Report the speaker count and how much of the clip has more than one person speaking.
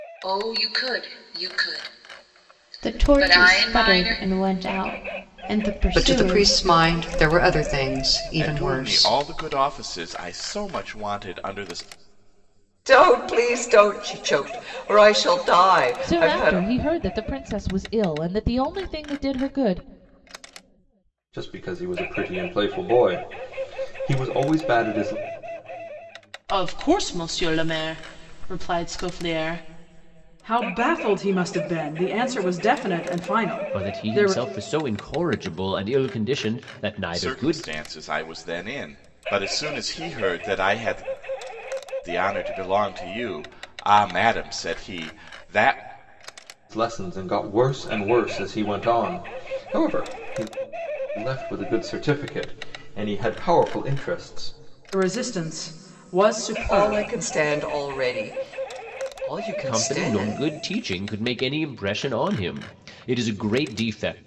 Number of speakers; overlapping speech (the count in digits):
10, about 10%